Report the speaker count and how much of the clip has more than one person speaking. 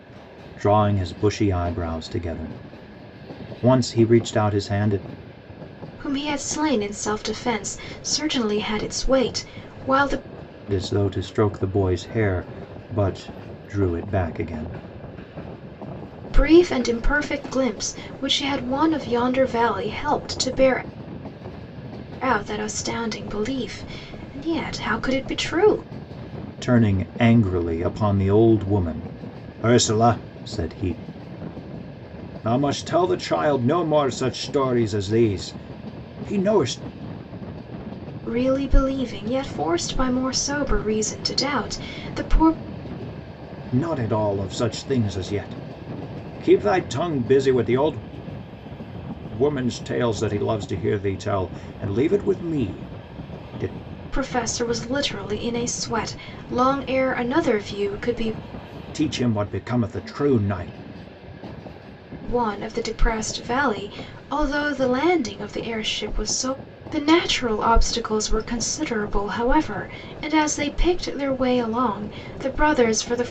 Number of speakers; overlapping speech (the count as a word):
two, no overlap